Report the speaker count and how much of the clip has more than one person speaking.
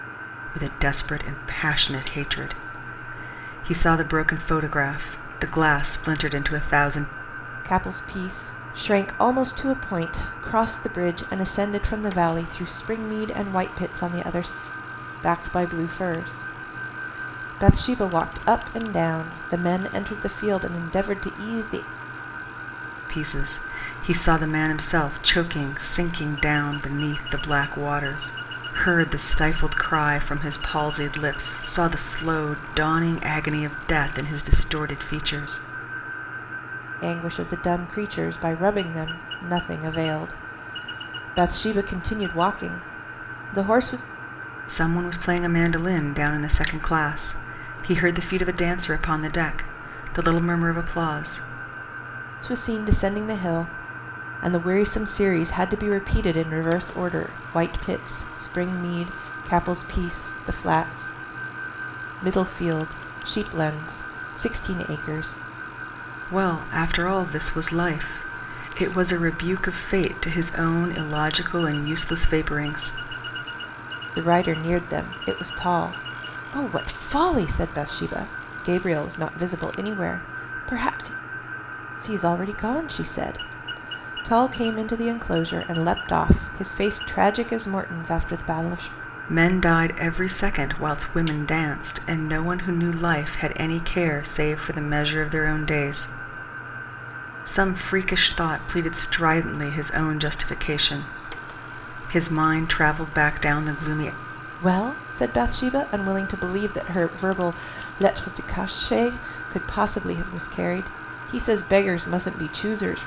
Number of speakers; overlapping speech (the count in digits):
2, no overlap